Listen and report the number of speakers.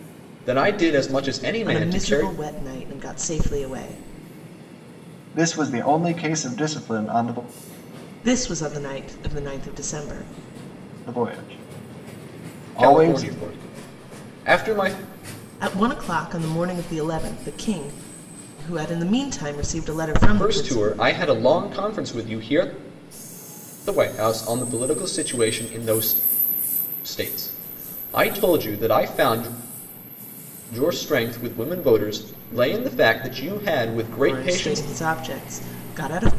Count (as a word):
three